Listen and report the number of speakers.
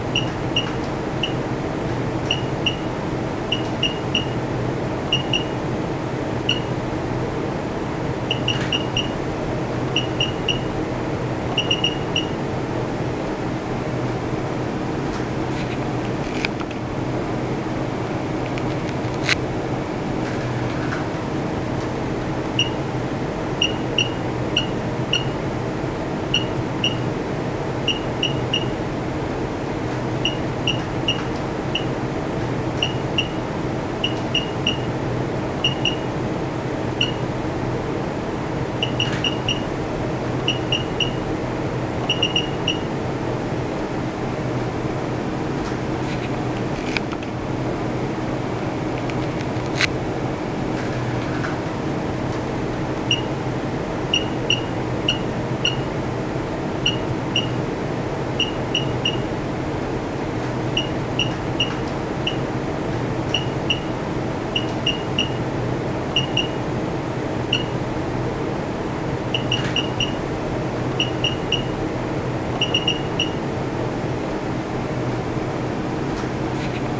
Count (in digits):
0